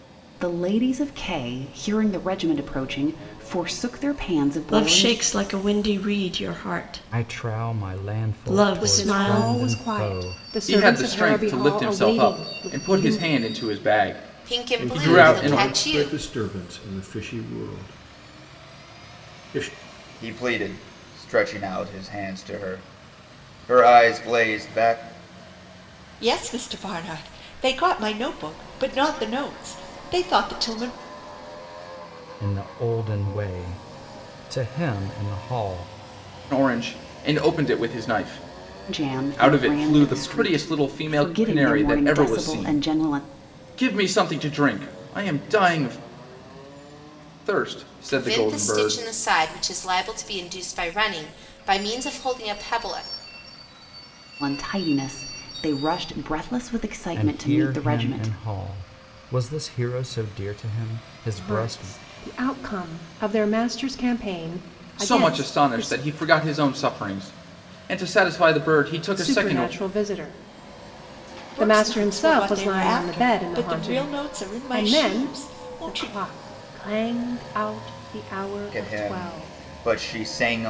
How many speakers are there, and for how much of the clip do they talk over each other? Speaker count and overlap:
9, about 27%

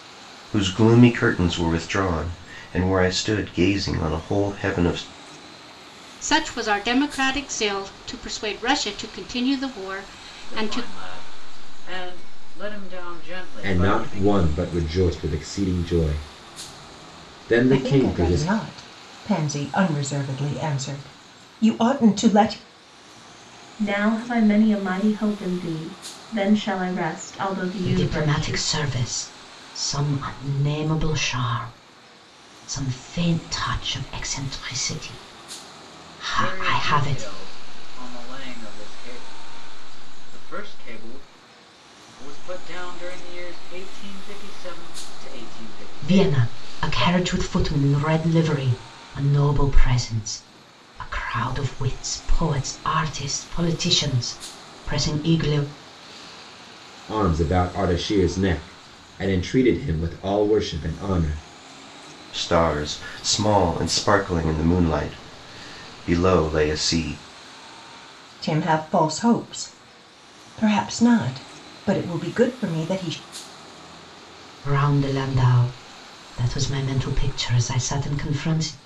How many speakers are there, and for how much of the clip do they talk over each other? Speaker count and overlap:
7, about 7%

